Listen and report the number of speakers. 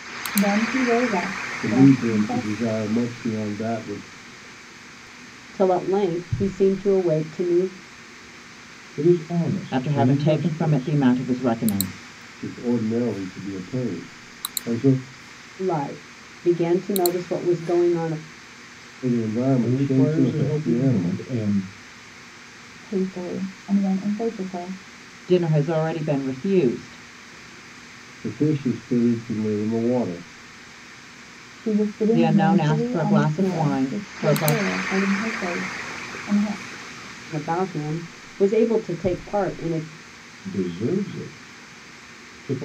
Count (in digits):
5